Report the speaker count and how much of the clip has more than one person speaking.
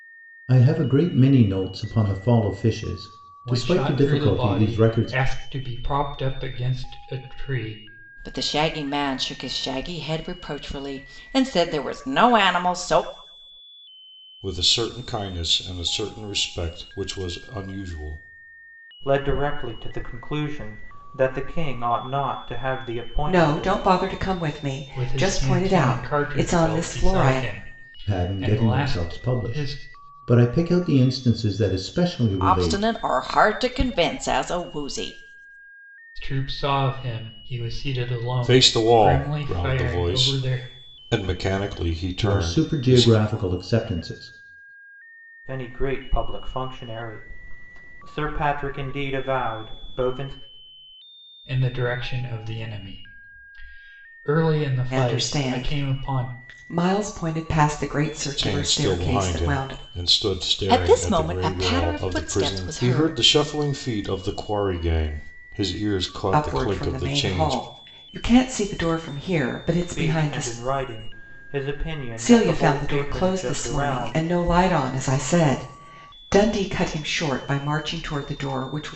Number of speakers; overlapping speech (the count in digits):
6, about 25%